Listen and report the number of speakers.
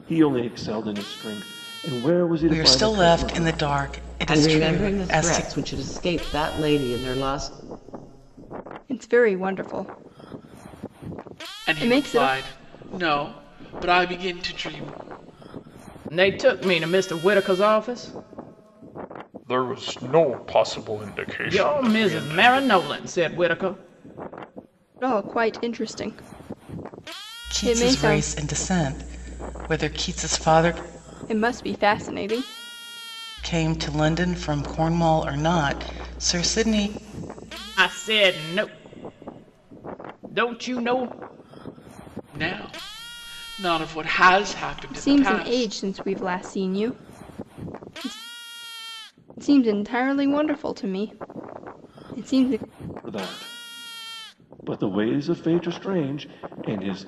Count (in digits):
7